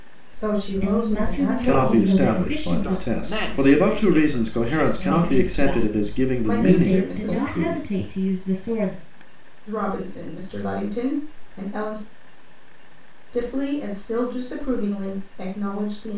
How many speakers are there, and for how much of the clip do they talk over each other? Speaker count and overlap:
4, about 44%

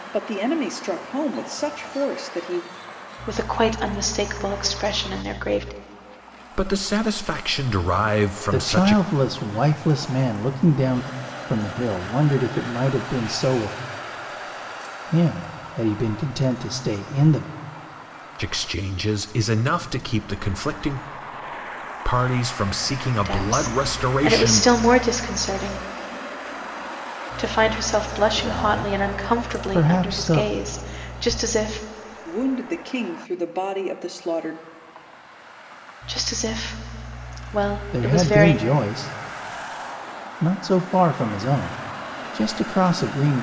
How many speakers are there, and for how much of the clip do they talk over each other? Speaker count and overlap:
4, about 11%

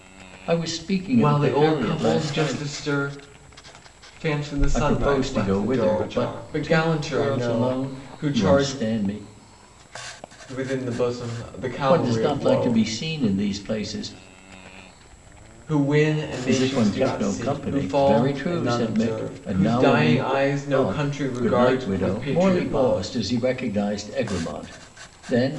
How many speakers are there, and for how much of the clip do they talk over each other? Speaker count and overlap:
2, about 49%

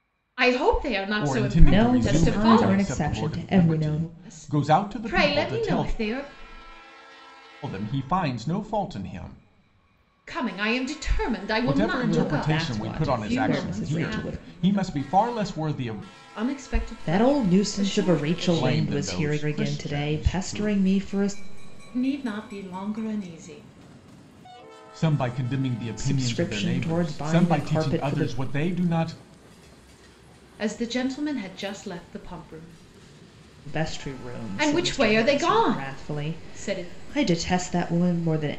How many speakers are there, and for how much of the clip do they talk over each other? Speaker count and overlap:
3, about 43%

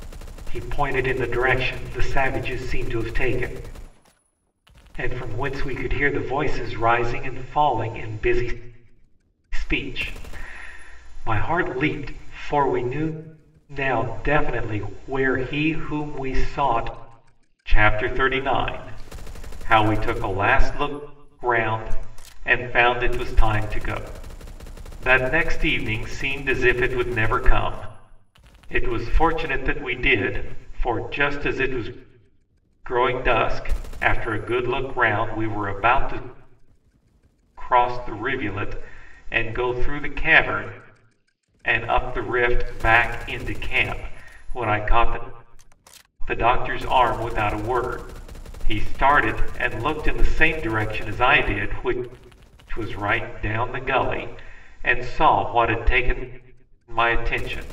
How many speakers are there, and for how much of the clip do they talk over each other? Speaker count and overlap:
1, no overlap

